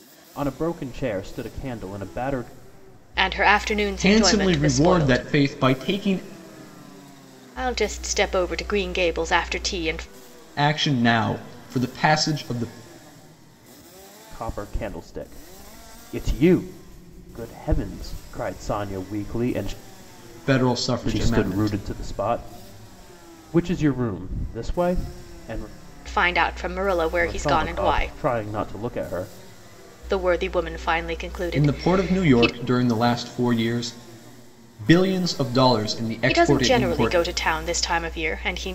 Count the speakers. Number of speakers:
three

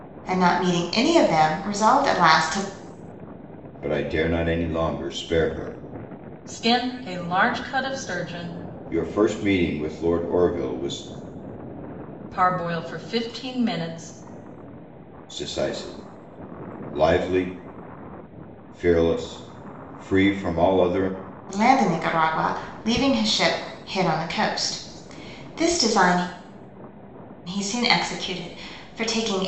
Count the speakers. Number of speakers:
three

